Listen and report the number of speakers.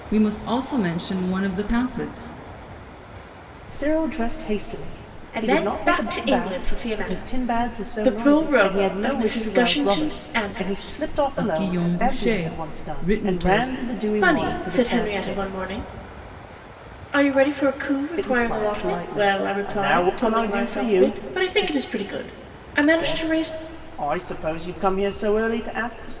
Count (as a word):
three